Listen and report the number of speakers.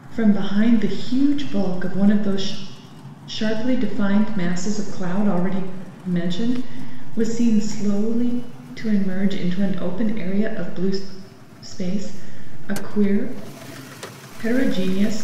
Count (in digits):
1